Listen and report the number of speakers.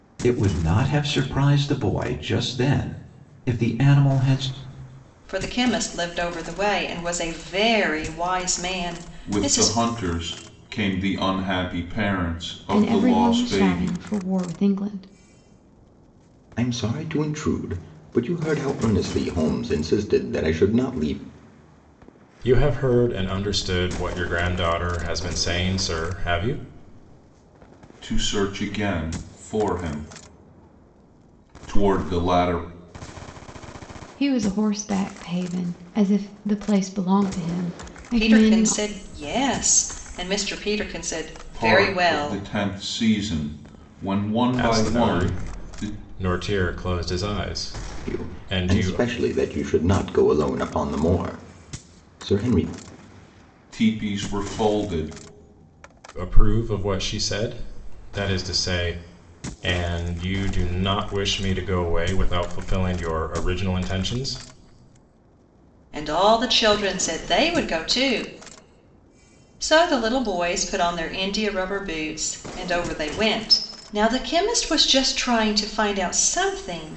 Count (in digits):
6